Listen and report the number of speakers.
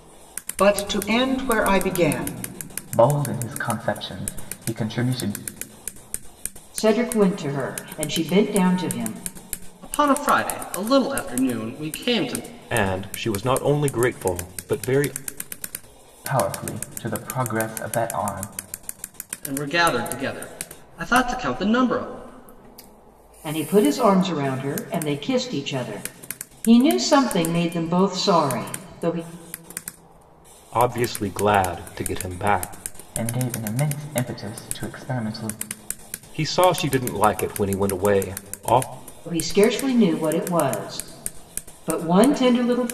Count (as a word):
five